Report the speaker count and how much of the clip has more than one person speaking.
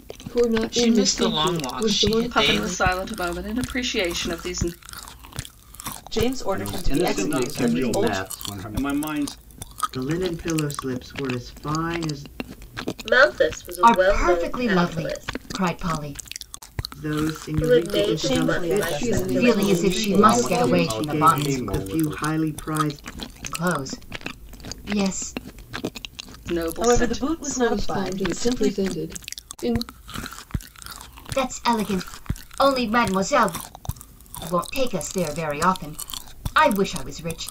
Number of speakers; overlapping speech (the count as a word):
nine, about 34%